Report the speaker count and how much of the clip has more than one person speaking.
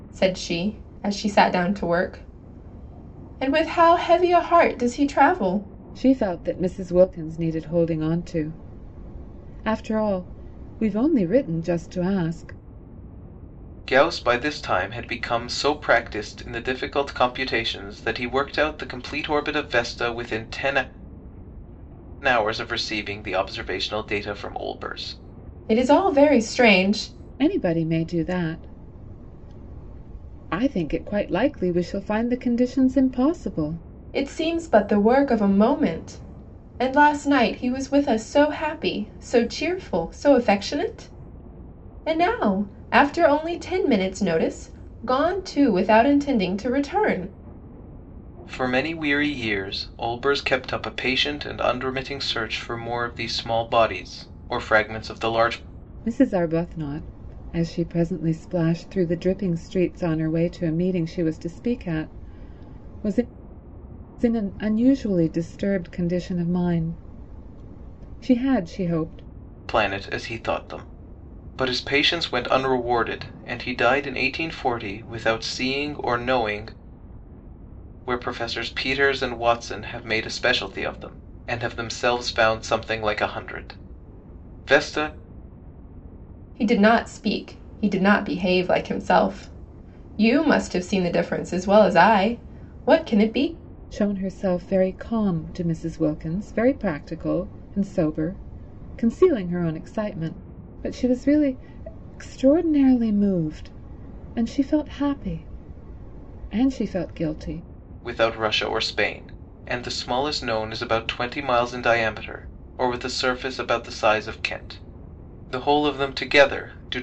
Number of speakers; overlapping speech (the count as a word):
three, no overlap